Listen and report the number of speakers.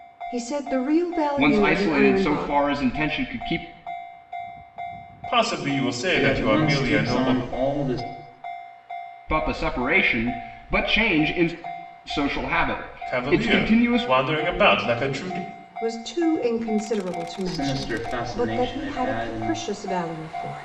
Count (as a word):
four